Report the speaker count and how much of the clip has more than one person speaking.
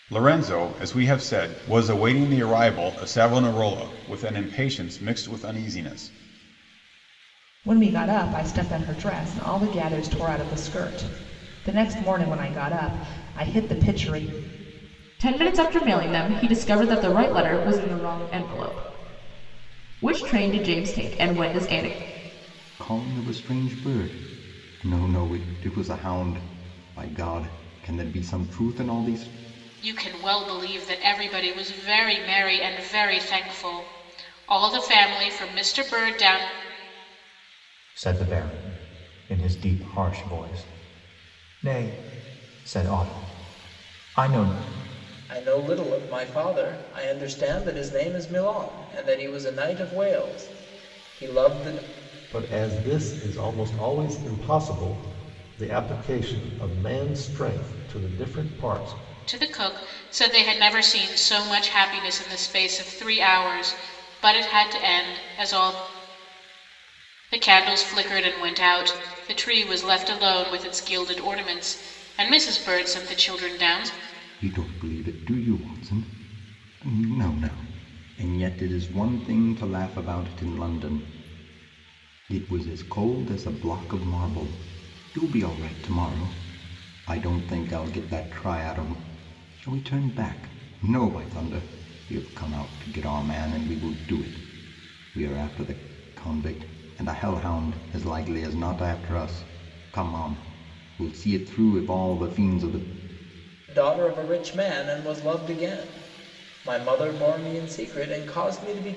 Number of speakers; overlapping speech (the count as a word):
eight, no overlap